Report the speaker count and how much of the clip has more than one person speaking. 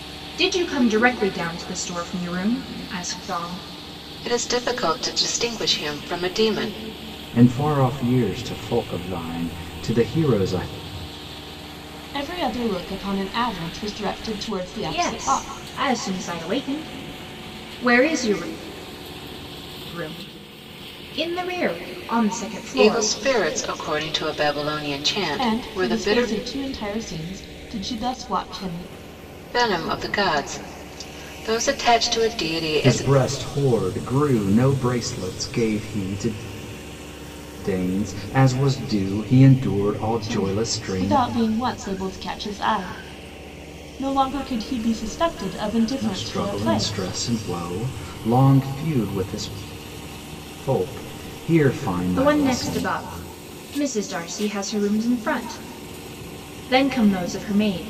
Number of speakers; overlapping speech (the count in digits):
4, about 9%